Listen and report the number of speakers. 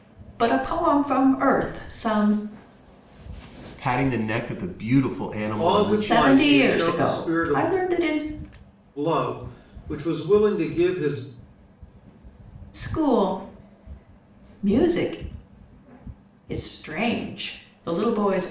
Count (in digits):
3